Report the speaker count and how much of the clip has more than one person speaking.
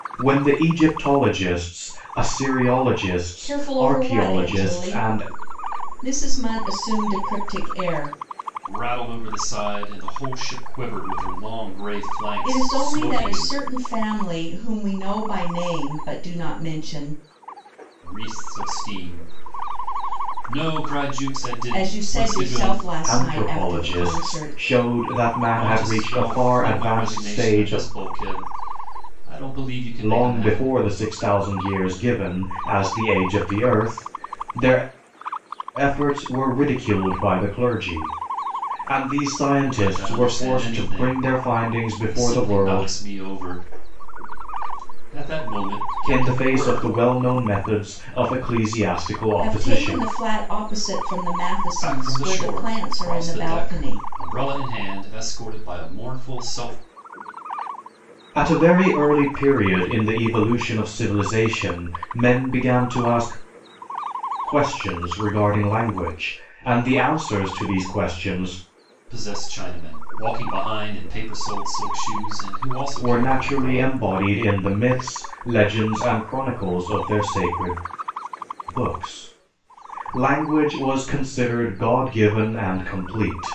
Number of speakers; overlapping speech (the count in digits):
3, about 19%